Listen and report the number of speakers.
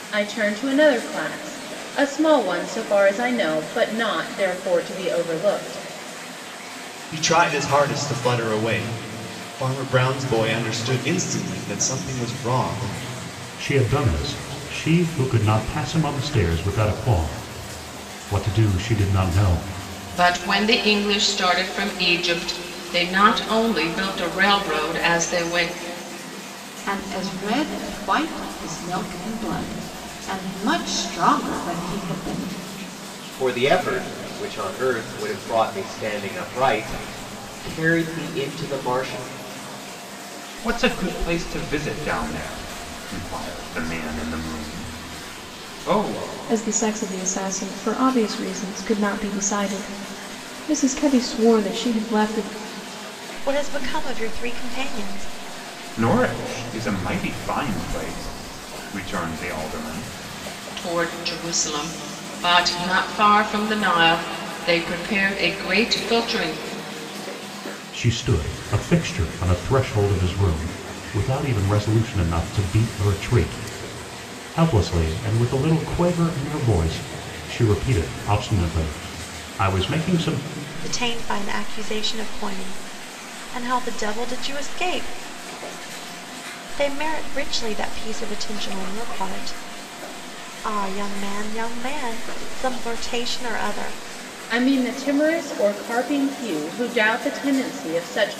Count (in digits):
9